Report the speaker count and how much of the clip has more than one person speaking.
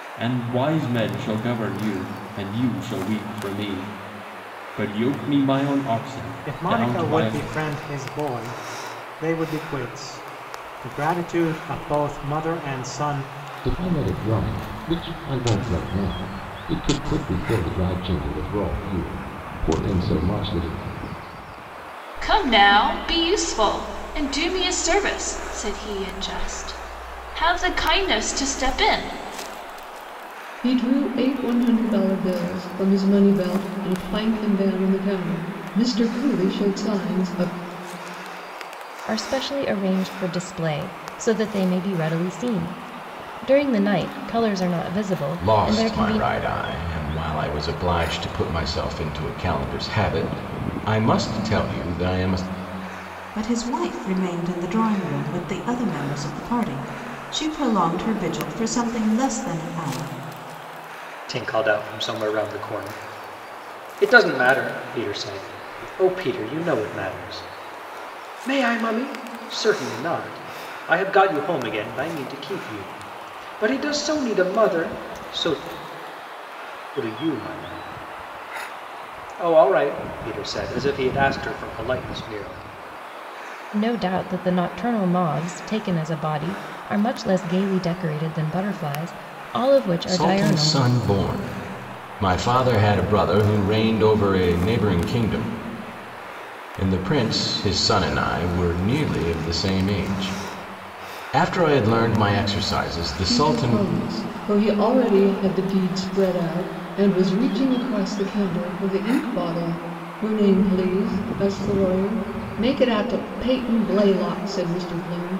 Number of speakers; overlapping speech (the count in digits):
9, about 3%